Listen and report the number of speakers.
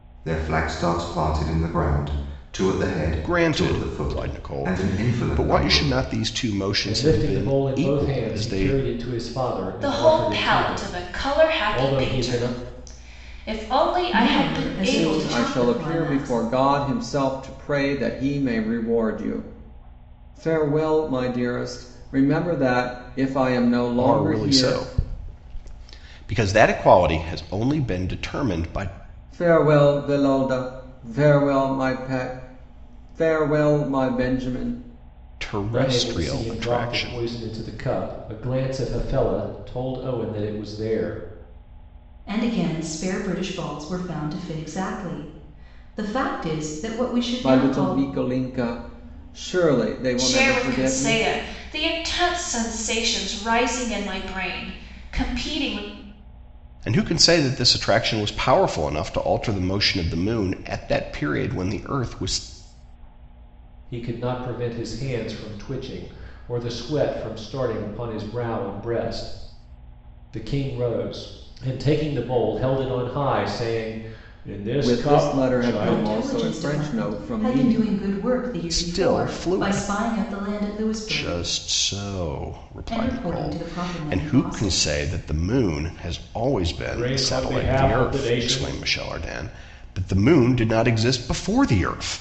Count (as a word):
six